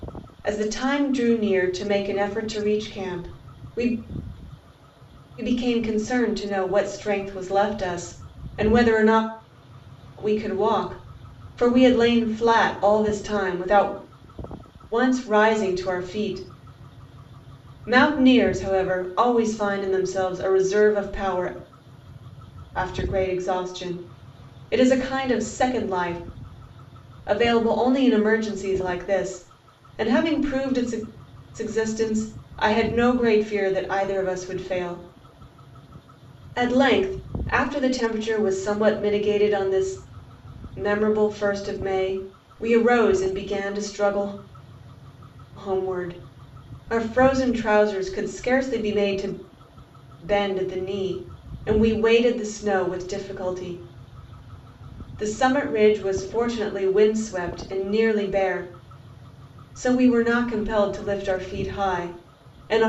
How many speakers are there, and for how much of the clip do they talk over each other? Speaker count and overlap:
1, no overlap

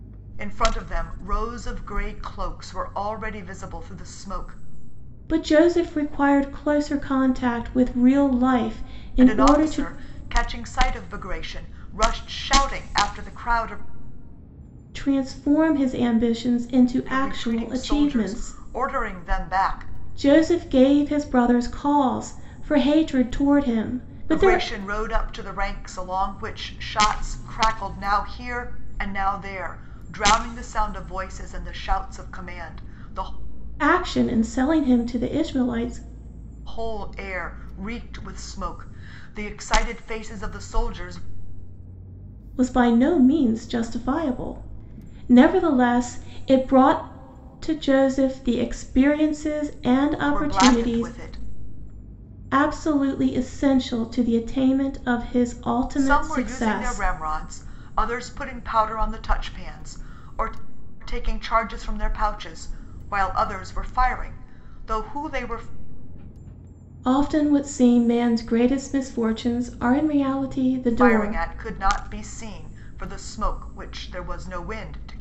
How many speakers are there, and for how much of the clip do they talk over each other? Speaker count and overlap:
2, about 7%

